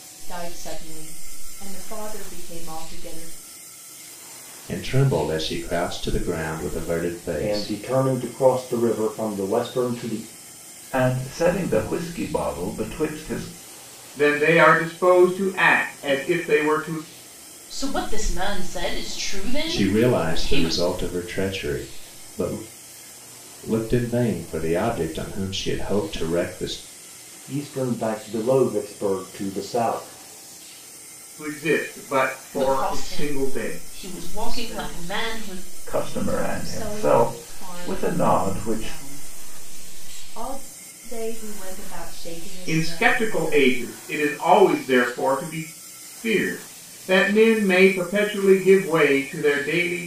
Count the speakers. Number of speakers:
6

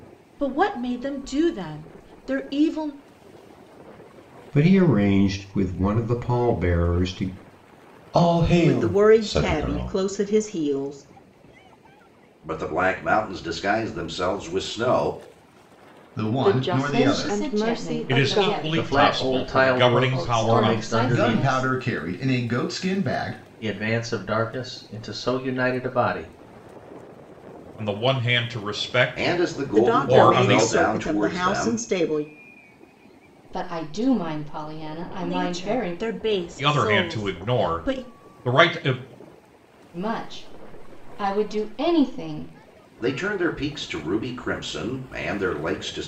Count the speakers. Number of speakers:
10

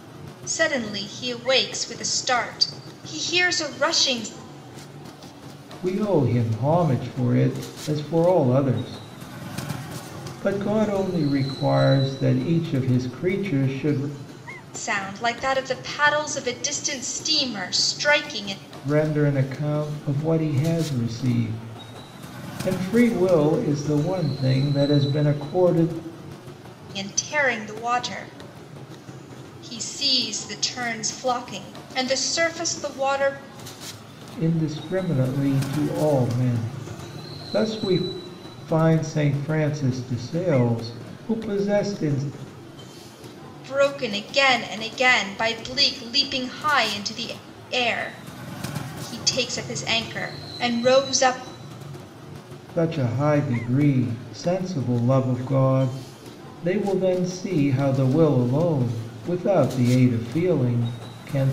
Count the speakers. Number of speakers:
2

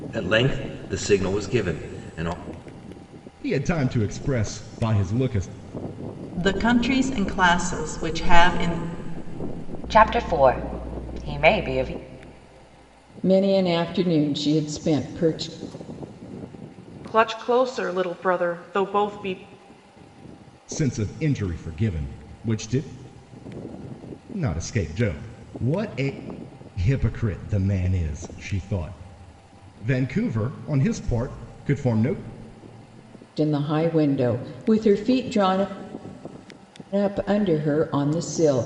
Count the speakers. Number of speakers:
6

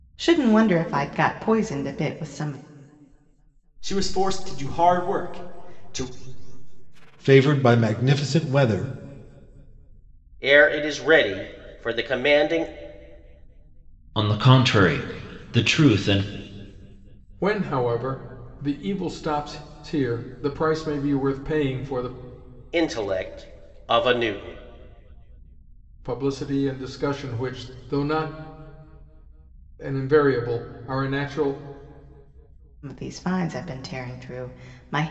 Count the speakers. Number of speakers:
6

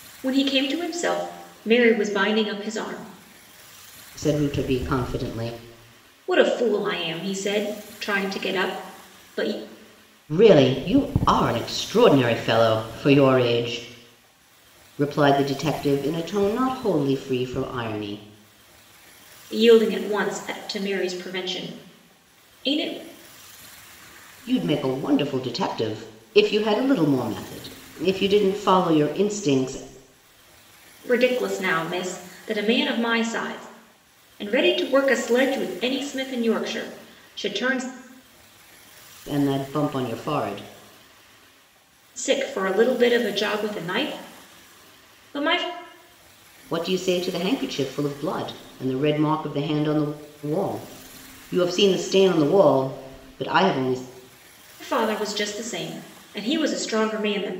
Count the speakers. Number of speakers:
2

